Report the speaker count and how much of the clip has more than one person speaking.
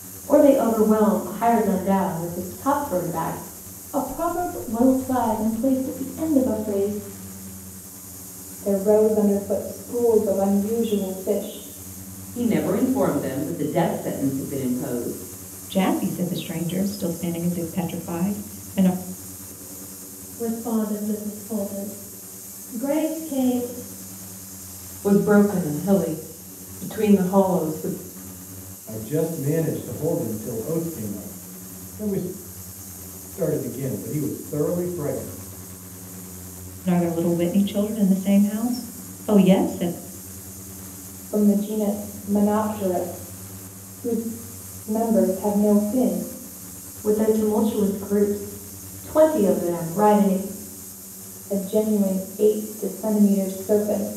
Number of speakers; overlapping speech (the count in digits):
8, no overlap